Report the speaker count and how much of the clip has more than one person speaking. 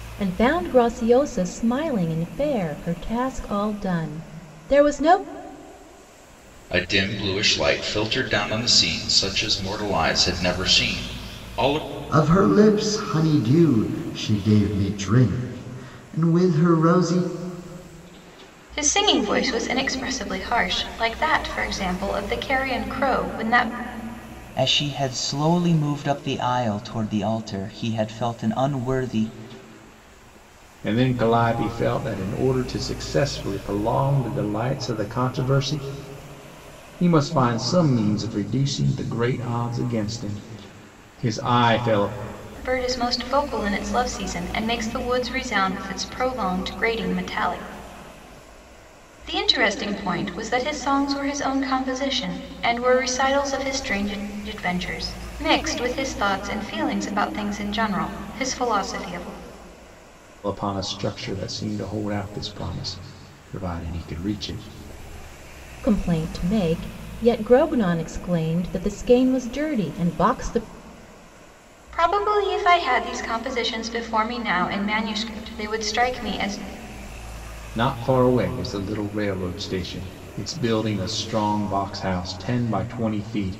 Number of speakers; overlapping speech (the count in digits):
6, no overlap